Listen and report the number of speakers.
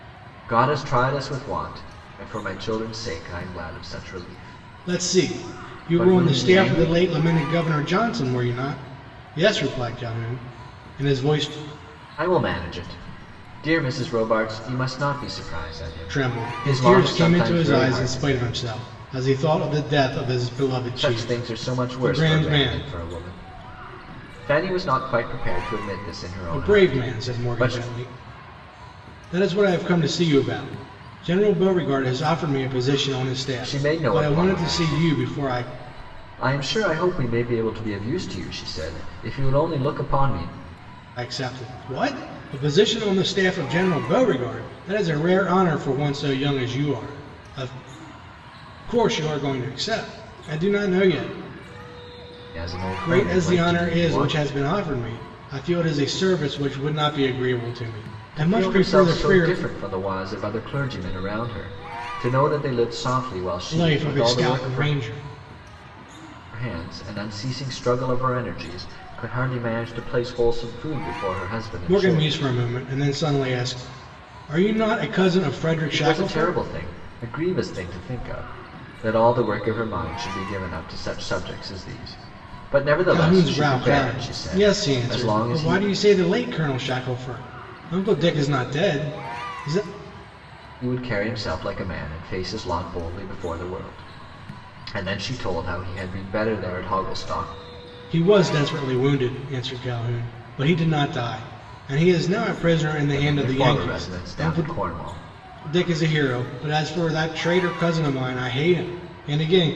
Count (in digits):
2